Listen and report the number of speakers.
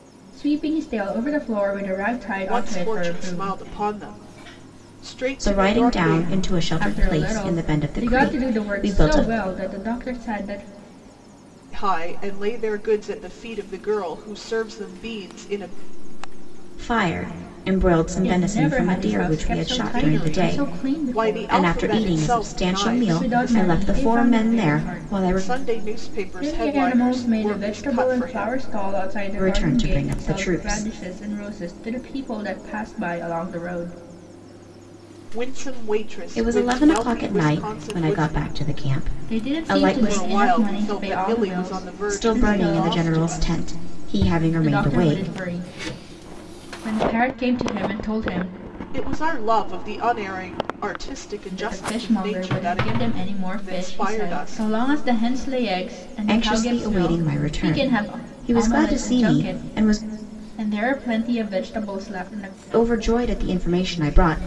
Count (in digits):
3